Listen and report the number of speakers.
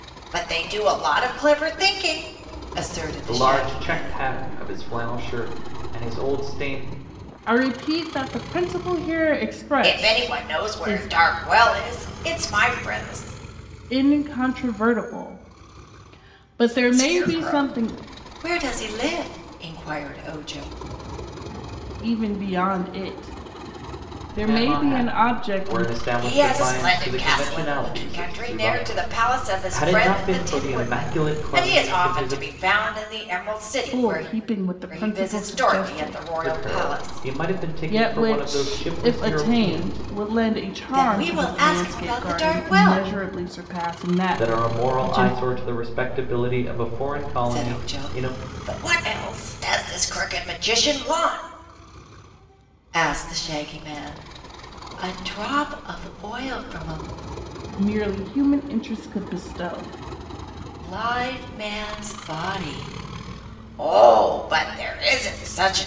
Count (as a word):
three